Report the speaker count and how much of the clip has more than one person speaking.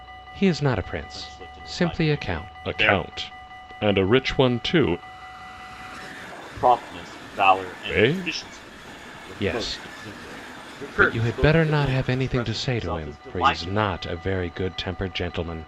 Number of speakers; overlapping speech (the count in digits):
2, about 42%